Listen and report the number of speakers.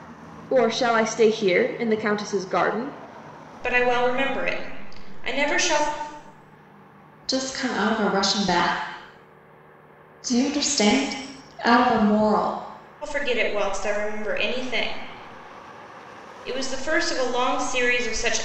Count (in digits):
3